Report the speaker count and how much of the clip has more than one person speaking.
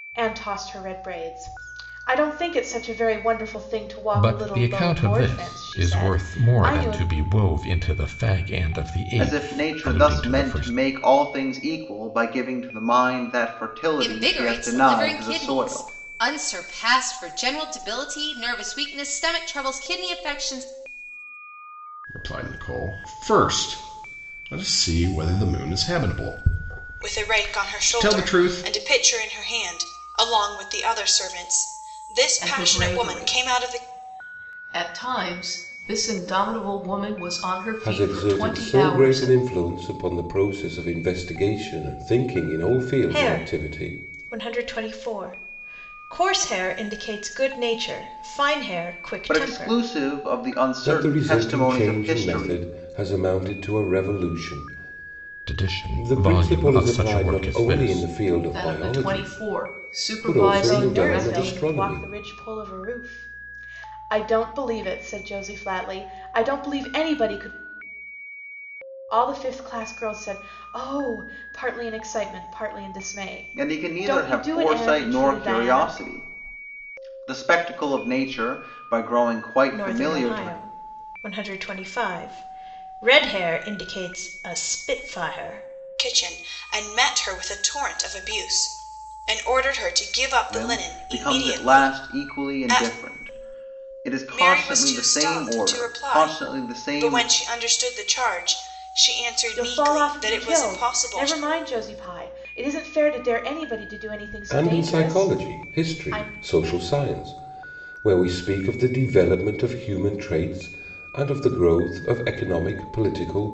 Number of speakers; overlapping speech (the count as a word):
nine, about 29%